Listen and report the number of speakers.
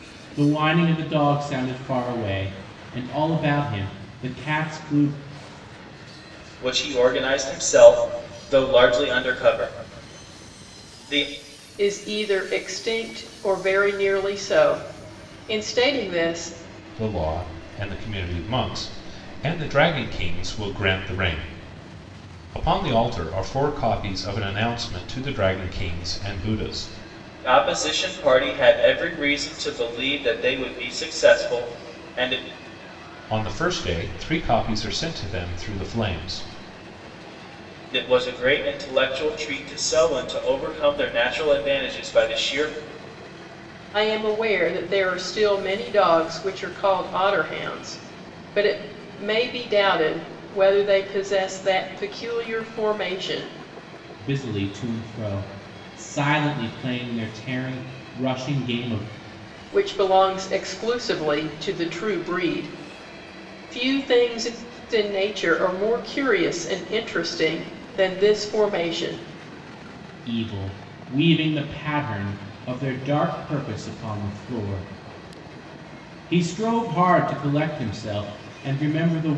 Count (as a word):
four